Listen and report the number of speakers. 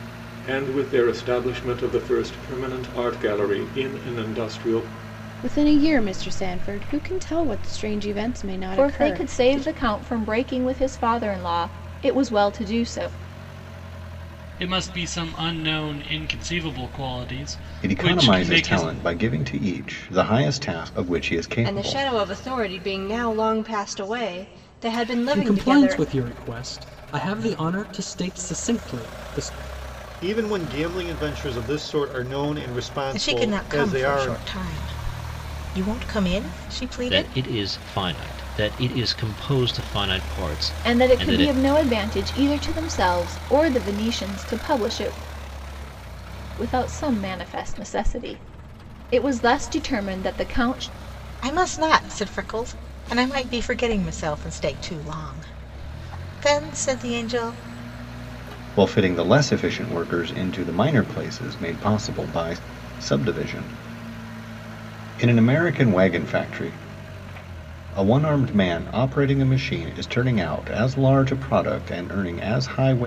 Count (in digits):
10